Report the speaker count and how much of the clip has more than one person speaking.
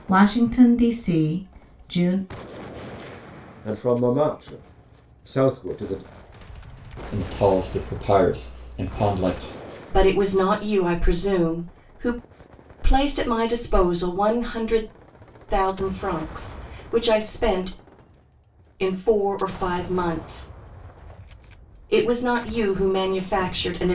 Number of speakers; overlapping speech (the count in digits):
4, no overlap